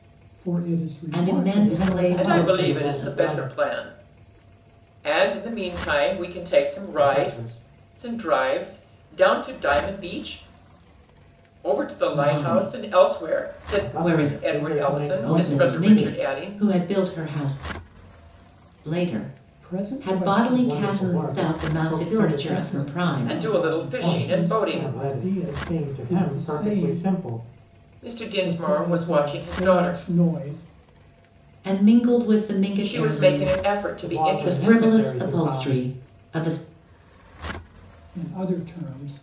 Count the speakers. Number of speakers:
four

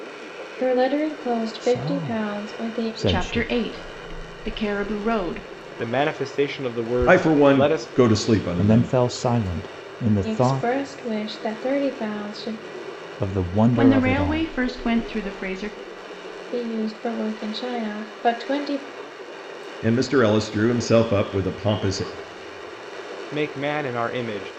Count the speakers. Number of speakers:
five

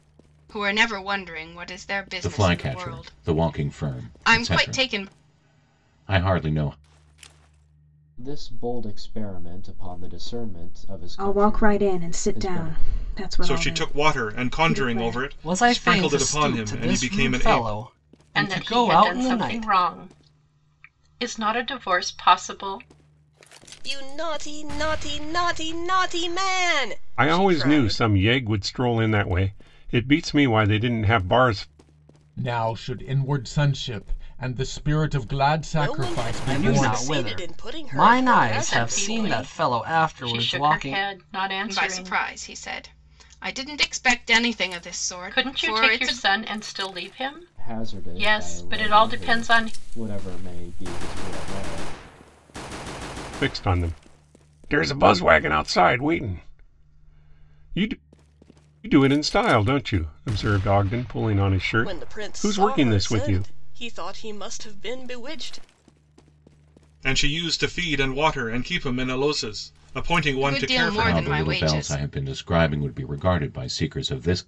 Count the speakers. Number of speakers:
ten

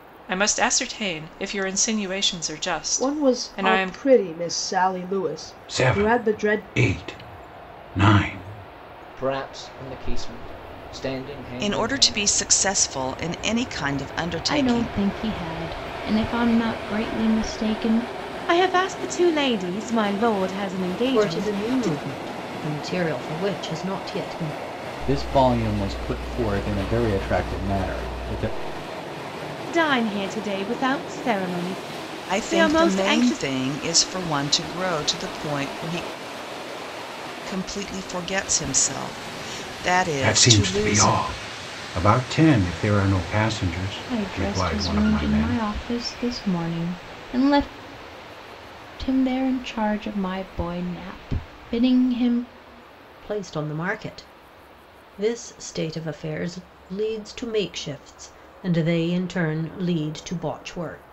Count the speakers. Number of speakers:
nine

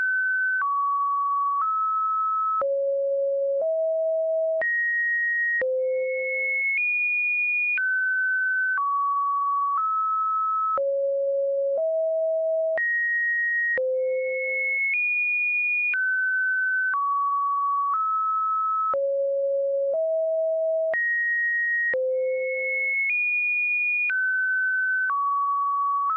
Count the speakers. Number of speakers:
zero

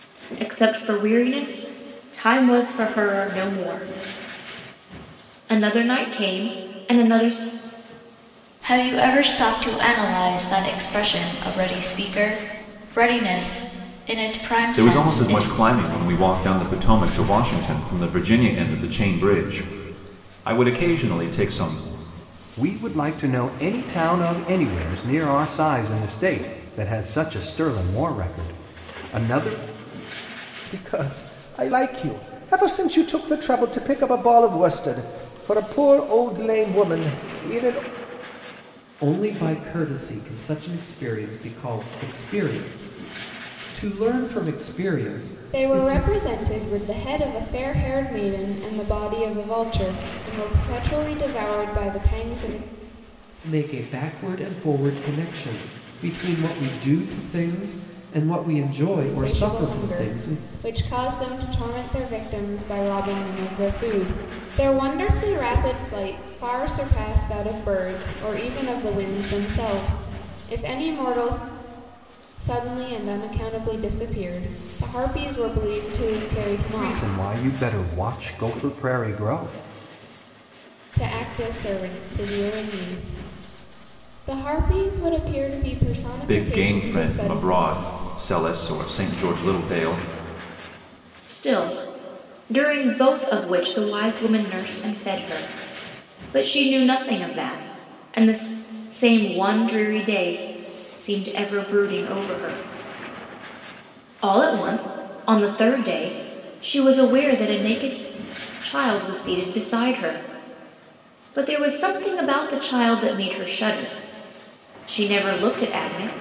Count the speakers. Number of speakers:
seven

